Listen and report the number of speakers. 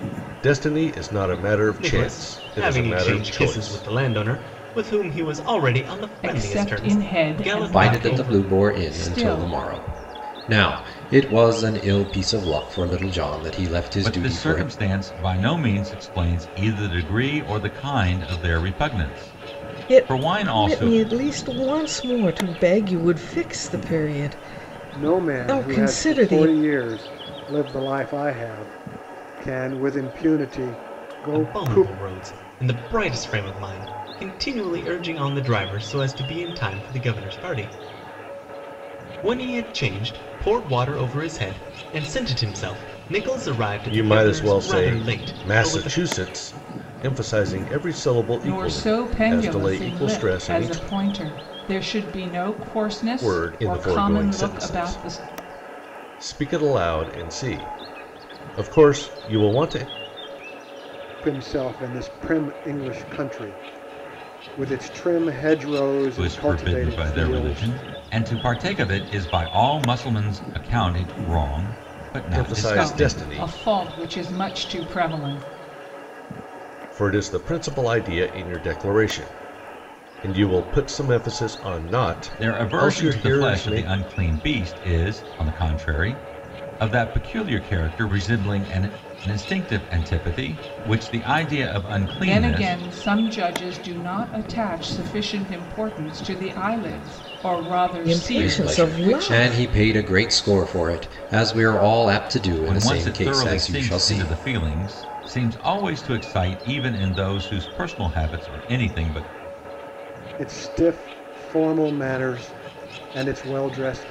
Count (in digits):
7